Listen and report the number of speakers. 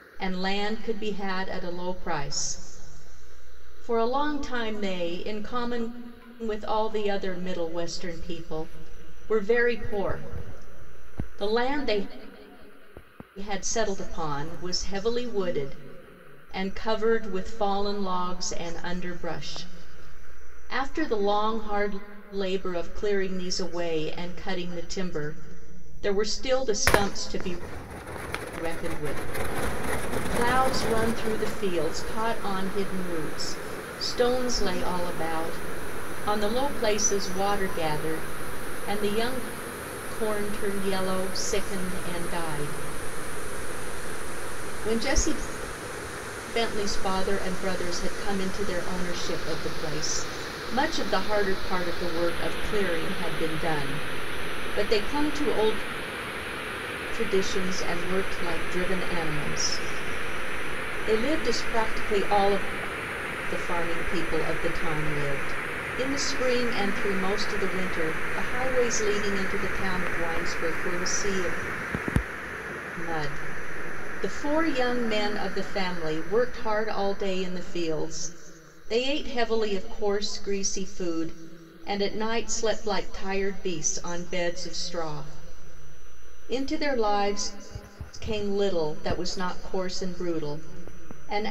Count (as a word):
one